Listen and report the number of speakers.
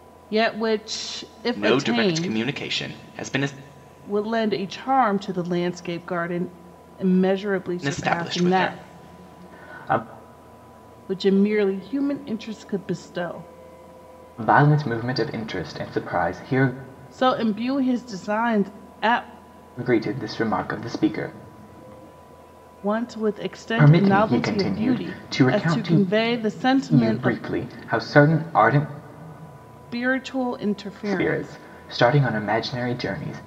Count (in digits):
2